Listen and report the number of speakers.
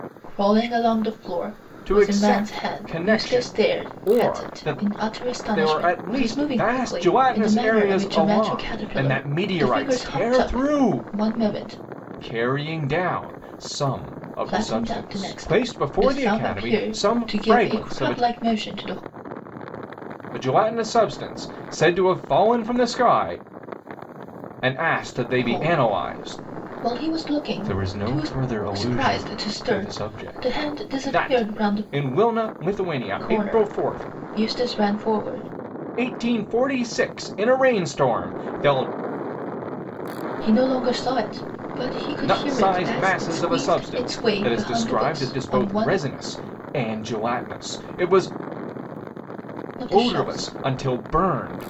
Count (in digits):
2